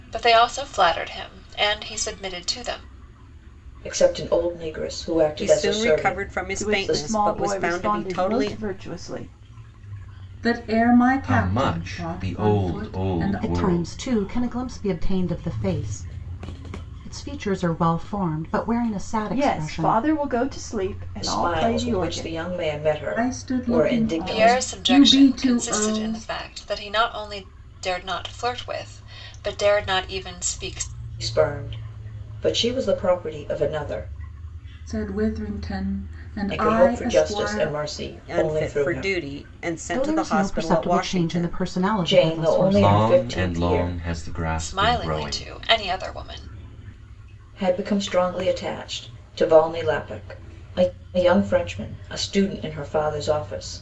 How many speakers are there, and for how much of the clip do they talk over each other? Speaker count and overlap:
seven, about 33%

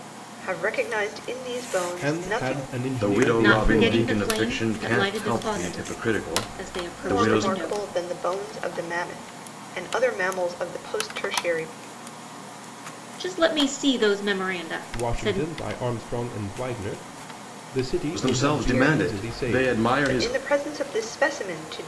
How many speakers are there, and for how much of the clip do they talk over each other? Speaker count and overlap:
four, about 35%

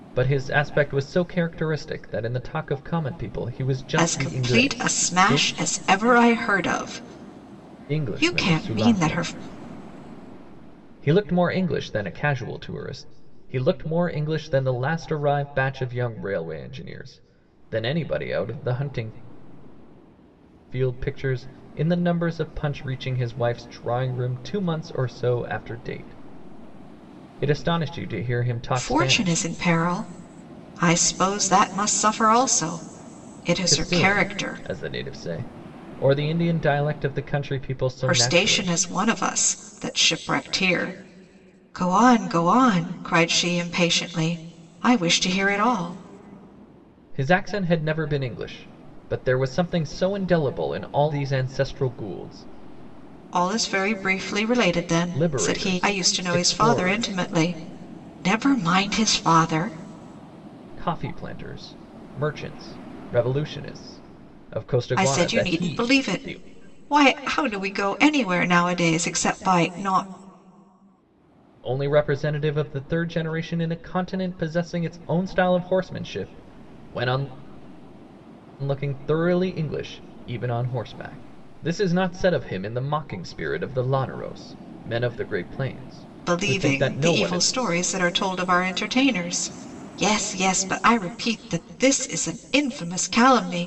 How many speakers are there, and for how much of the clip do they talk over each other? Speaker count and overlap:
two, about 11%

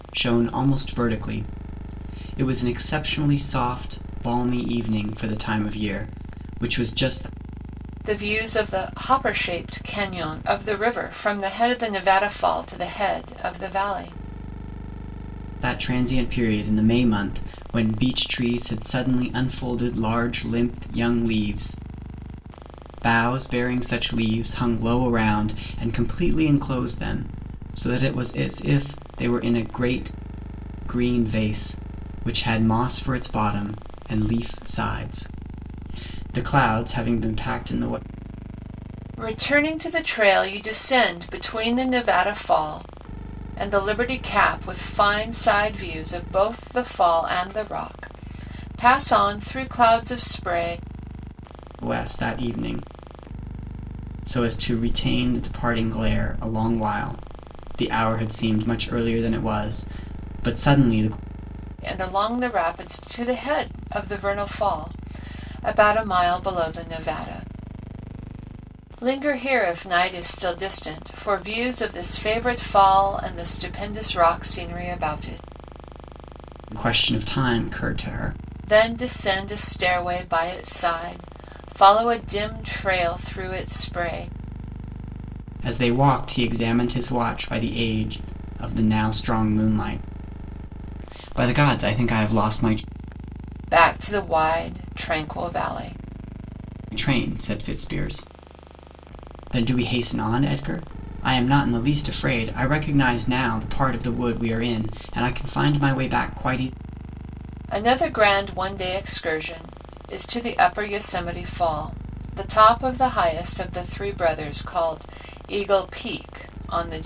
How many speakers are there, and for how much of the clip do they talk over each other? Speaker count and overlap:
two, no overlap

